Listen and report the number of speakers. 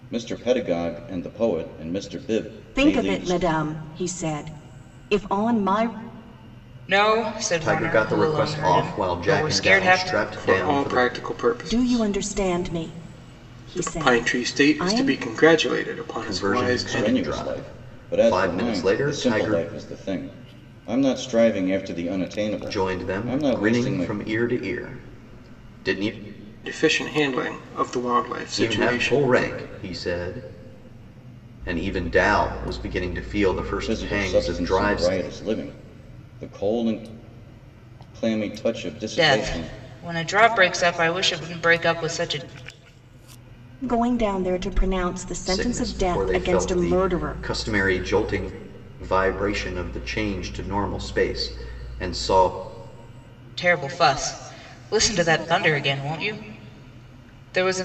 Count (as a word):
five